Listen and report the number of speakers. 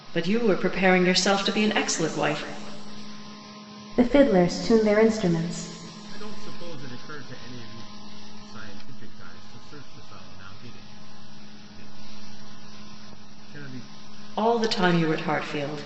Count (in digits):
3